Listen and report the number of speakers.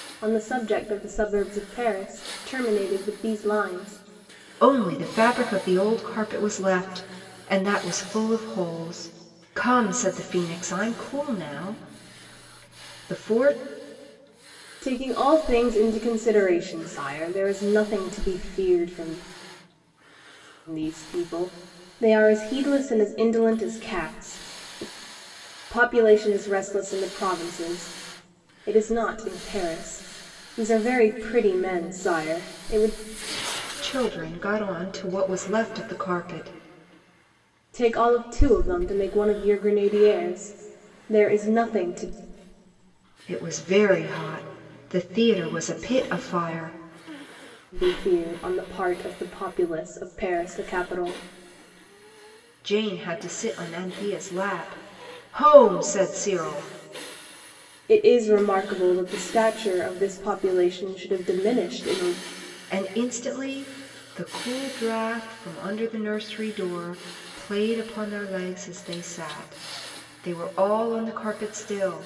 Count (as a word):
two